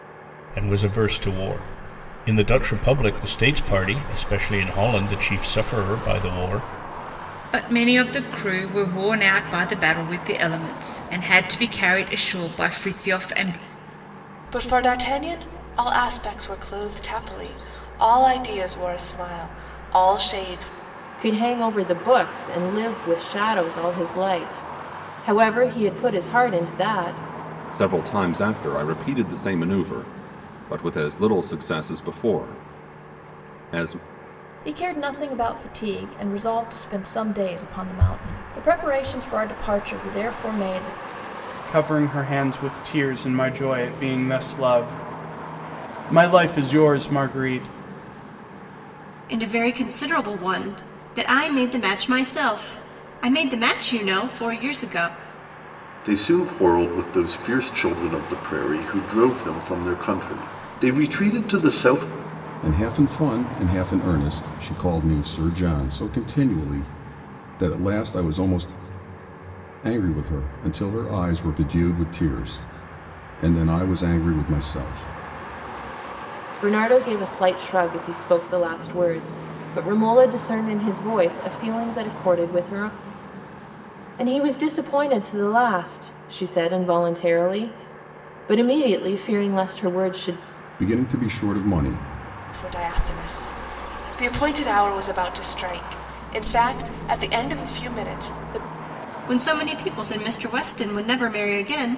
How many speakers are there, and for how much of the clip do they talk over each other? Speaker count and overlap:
10, no overlap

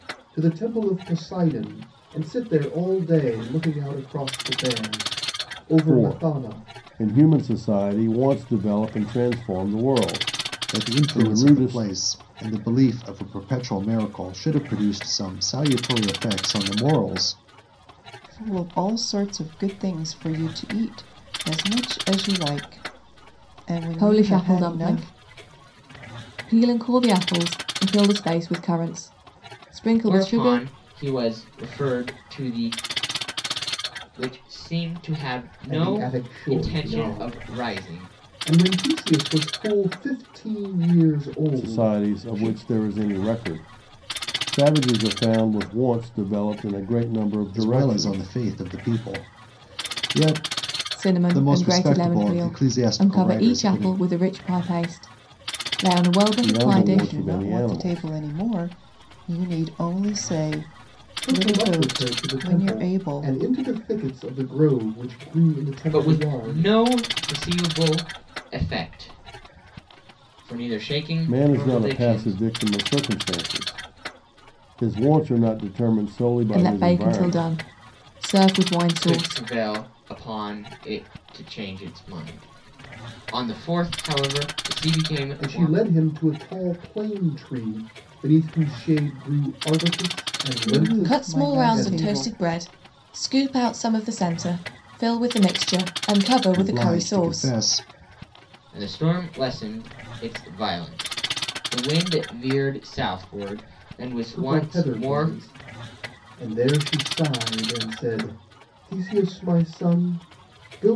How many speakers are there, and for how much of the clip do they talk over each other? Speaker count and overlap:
6, about 21%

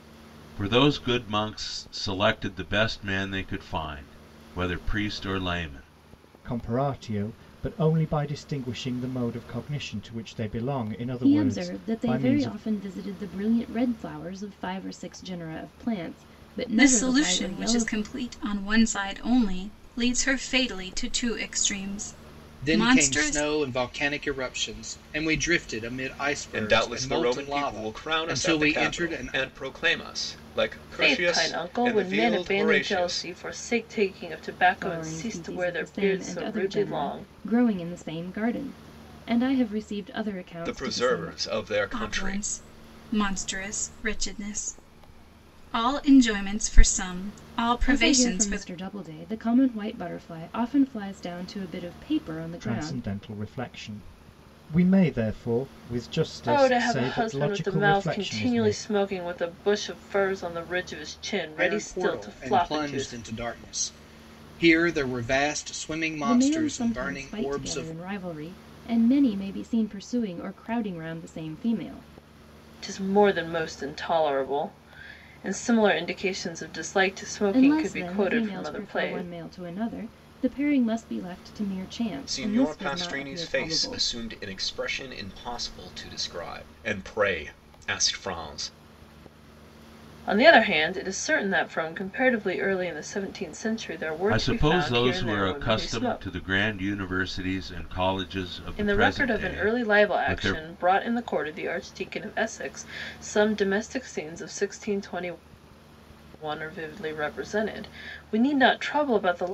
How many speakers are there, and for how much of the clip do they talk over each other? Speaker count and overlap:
7, about 25%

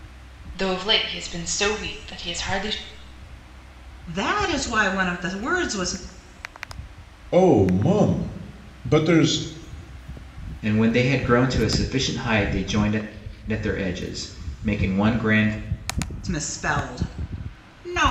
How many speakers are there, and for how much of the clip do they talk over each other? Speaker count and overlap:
4, no overlap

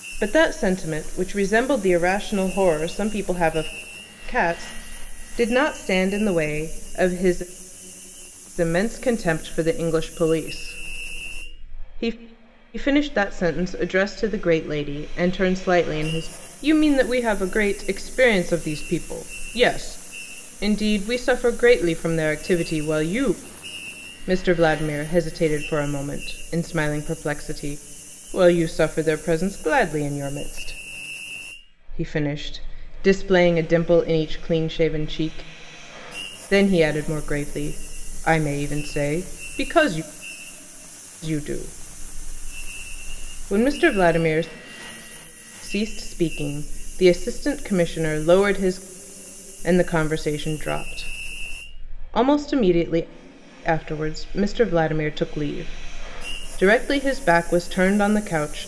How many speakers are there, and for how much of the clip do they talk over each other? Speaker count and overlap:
1, no overlap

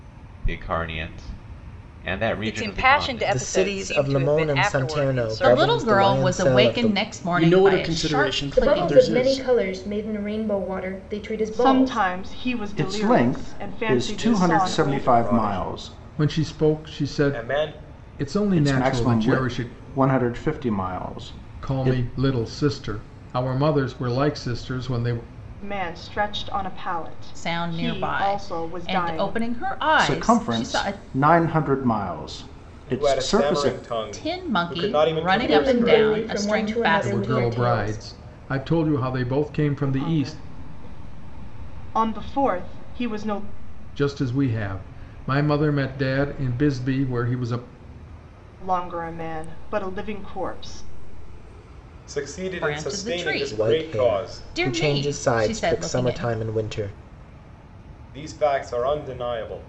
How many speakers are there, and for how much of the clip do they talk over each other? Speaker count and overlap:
10, about 44%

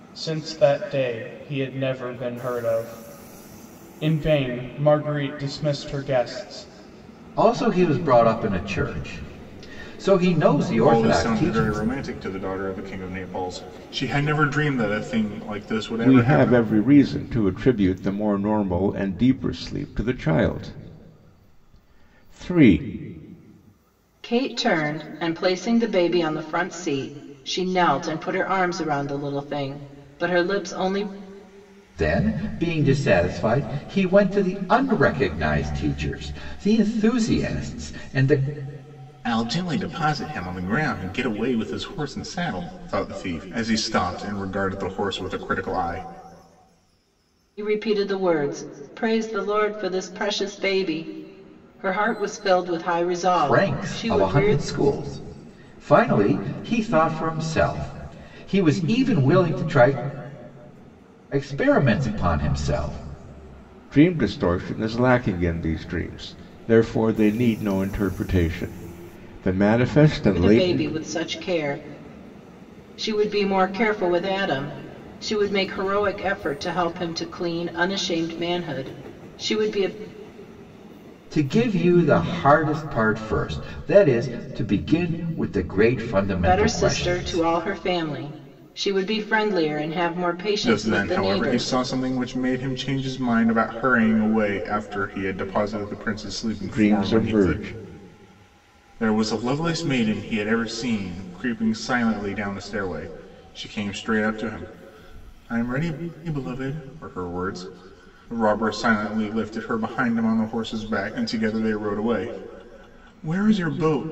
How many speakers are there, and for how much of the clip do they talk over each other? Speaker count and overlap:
5, about 6%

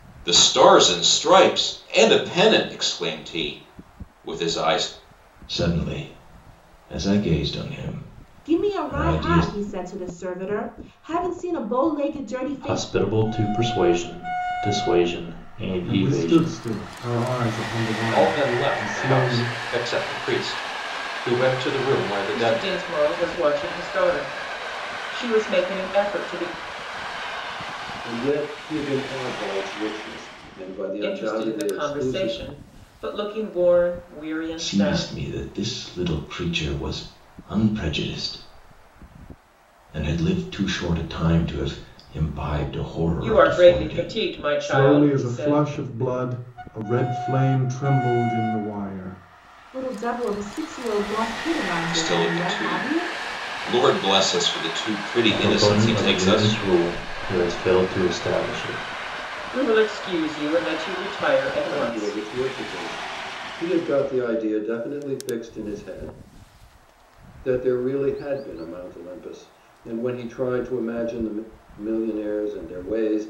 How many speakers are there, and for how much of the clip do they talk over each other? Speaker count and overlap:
8, about 15%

